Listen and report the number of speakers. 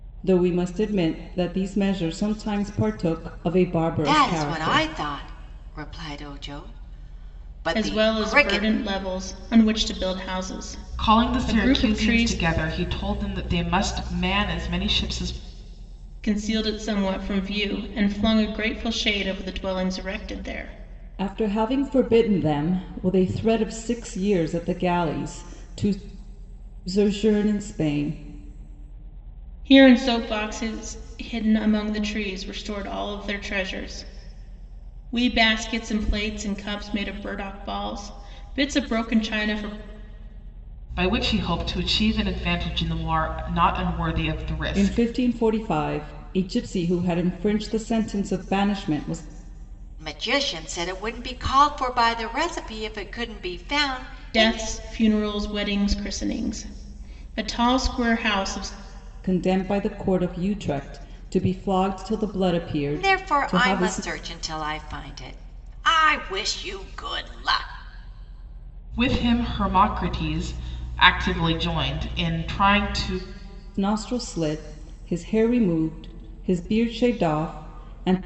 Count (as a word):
four